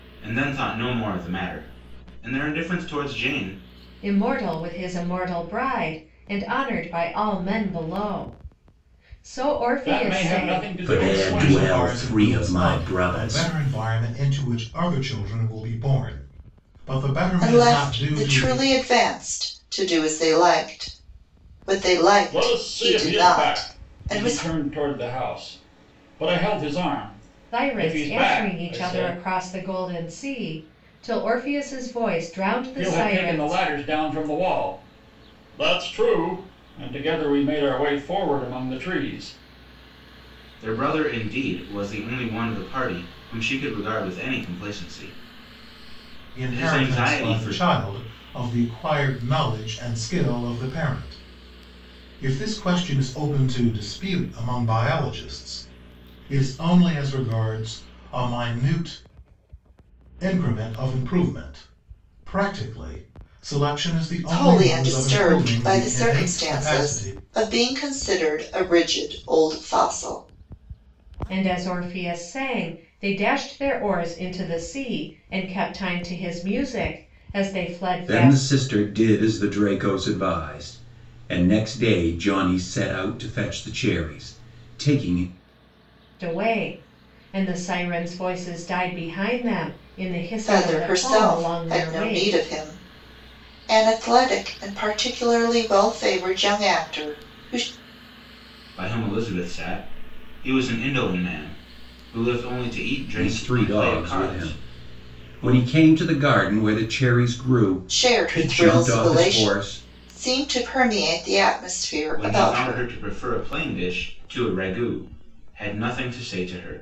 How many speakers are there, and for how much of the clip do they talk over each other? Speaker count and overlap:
six, about 19%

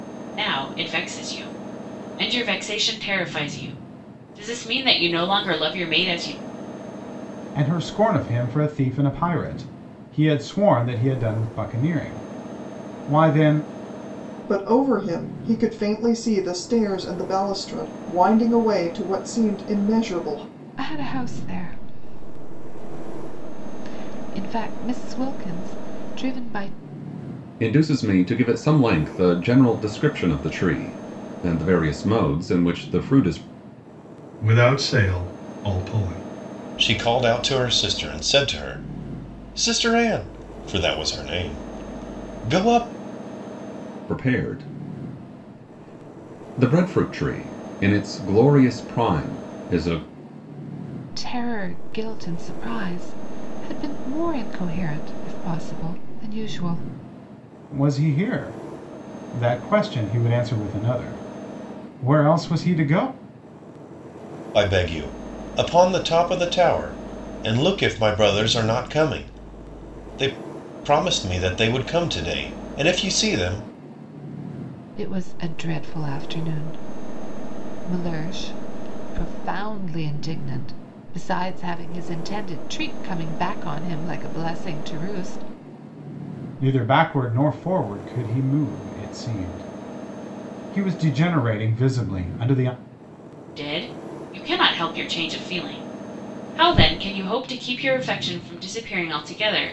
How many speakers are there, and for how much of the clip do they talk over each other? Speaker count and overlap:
seven, no overlap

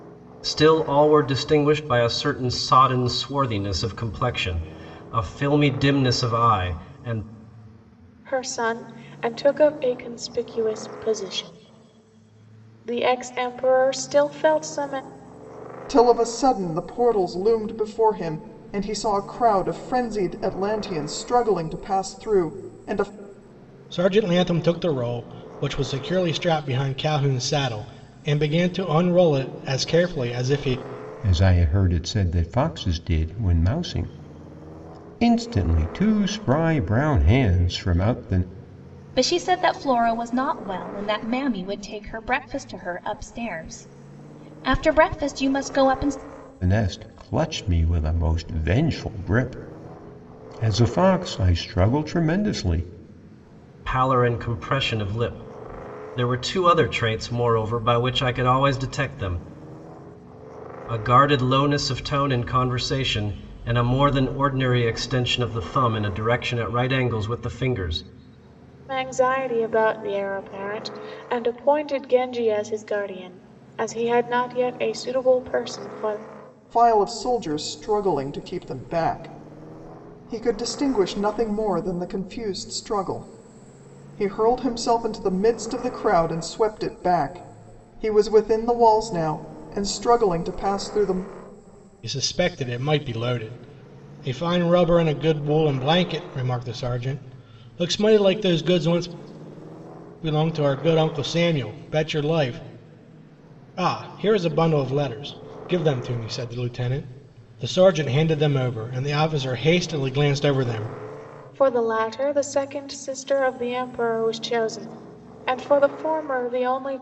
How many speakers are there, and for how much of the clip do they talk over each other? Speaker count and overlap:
six, no overlap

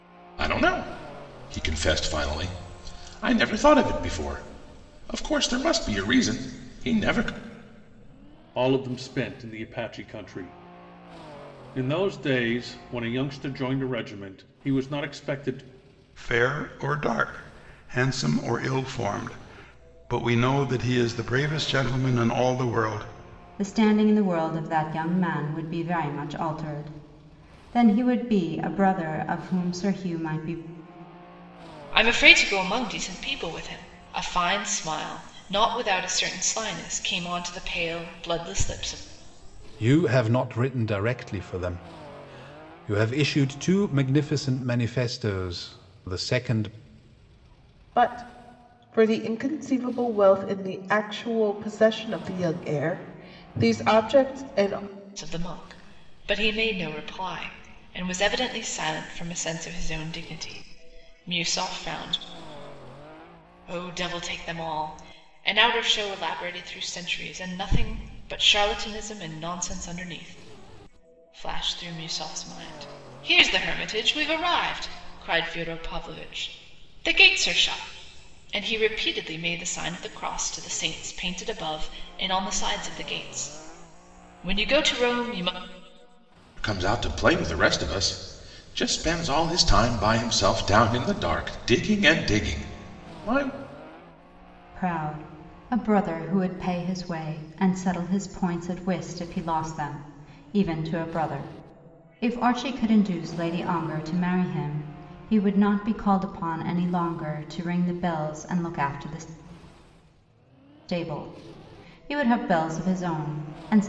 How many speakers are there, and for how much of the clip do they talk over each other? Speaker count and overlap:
seven, no overlap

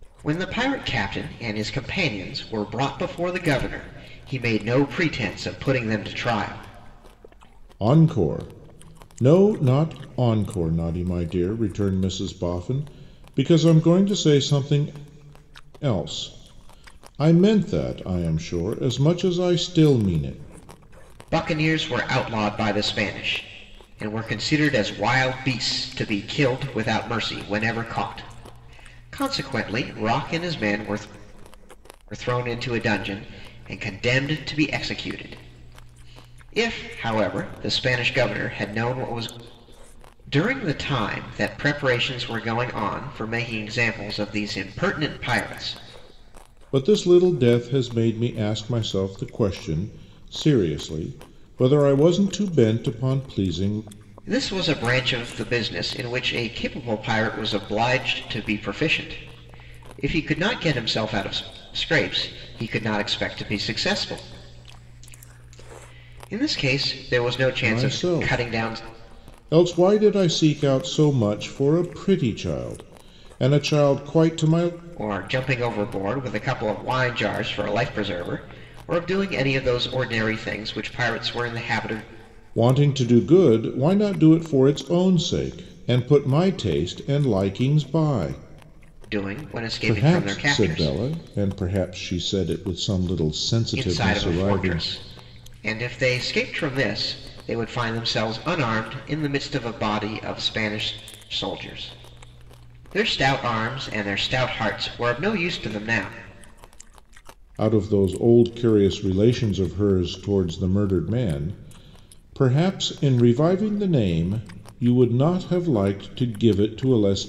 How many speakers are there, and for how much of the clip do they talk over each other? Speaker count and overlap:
two, about 3%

